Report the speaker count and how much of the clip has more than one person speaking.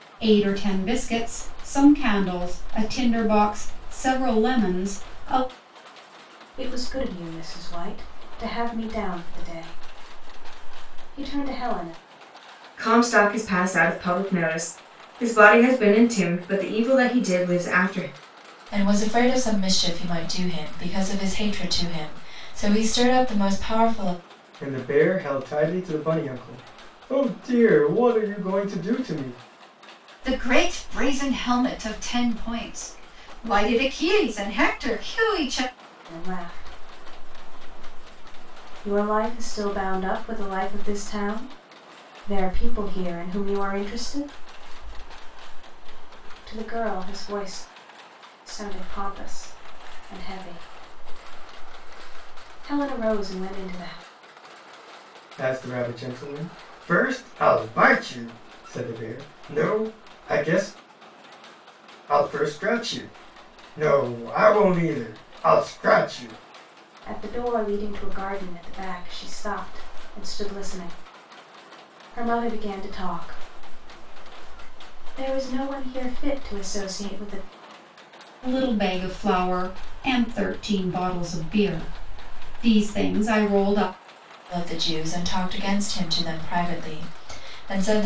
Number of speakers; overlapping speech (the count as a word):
six, no overlap